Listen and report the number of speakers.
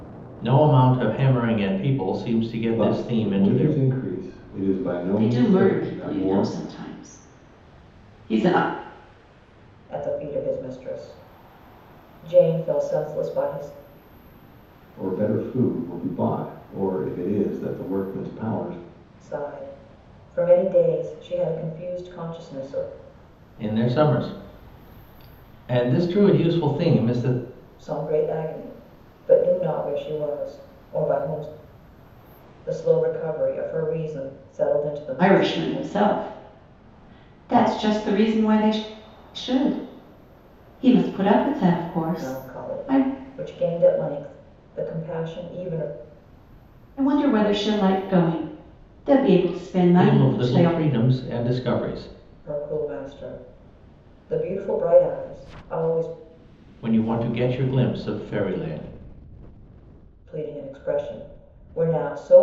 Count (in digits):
4